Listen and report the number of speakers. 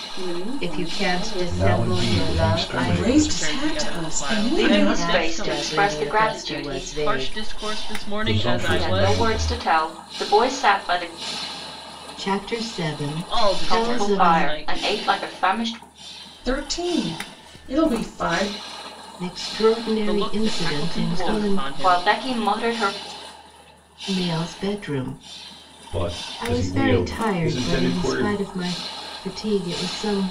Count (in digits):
6